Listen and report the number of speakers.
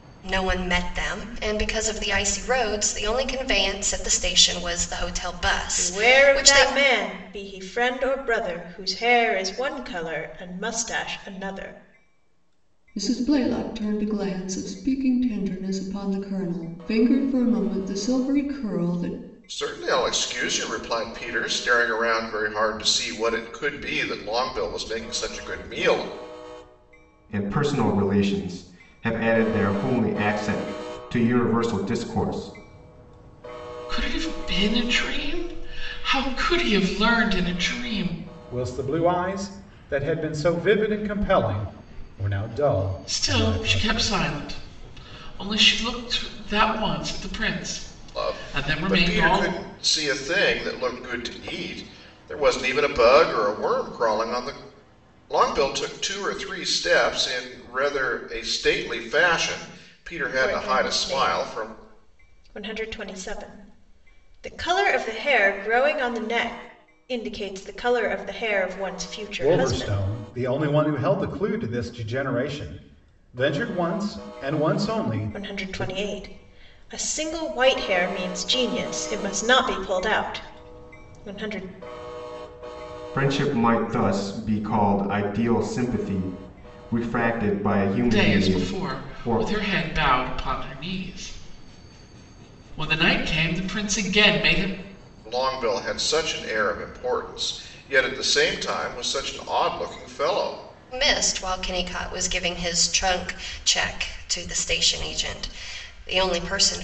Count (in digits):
7